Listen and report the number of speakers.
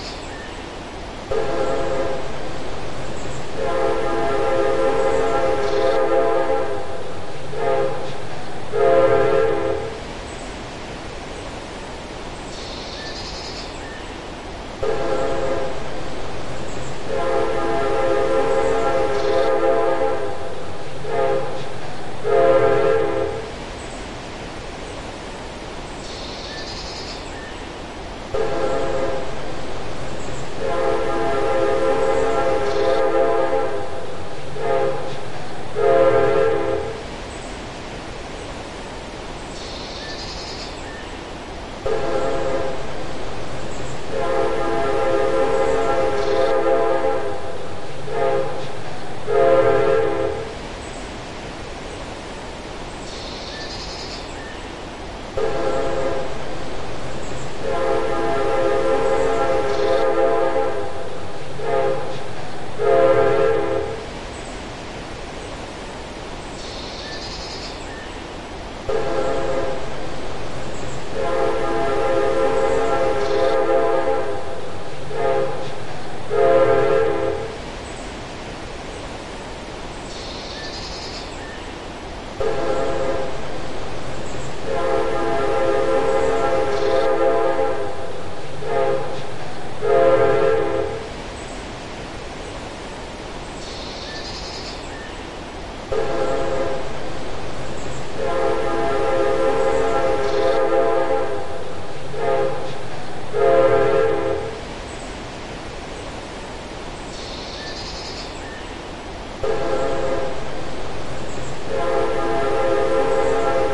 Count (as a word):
zero